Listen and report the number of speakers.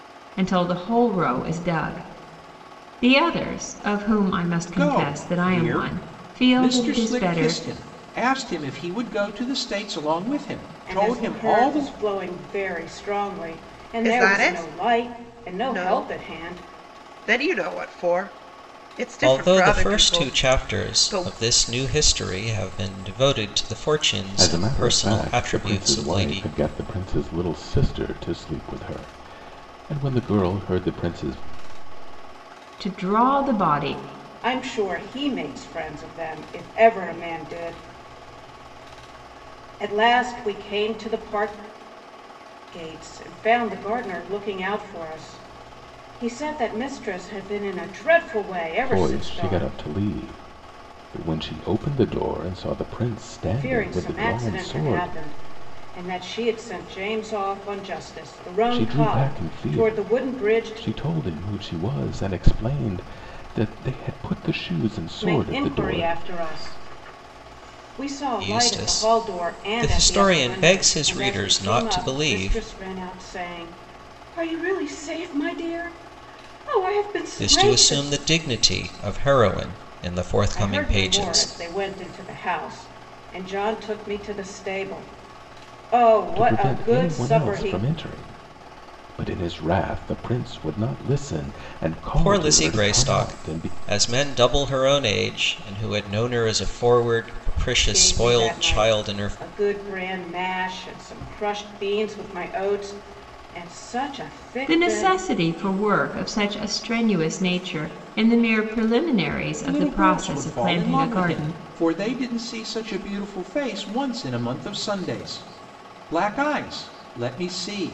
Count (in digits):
6